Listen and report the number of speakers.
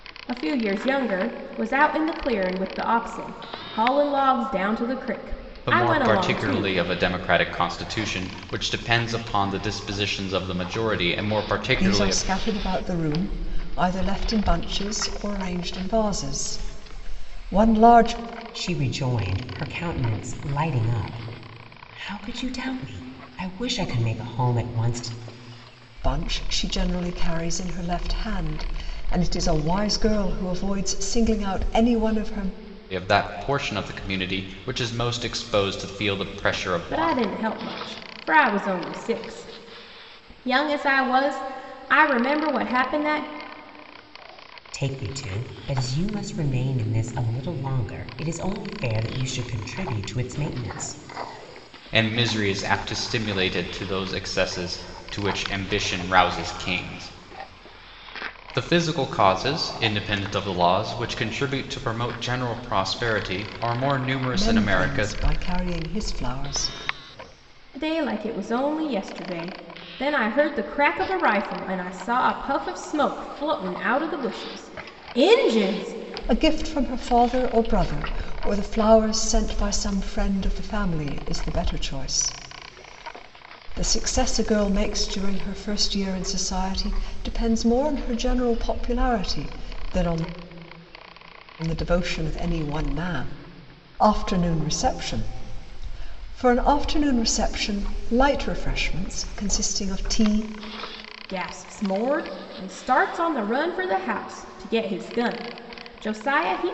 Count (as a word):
four